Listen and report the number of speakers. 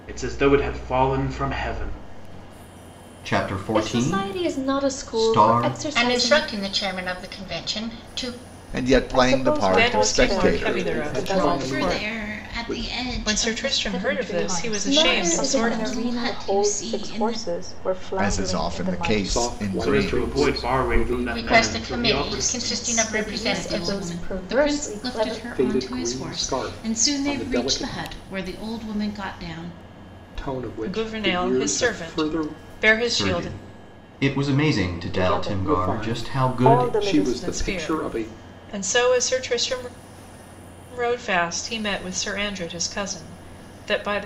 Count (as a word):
nine